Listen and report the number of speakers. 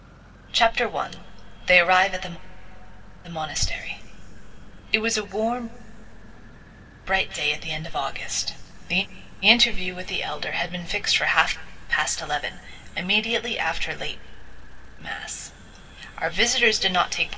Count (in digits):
1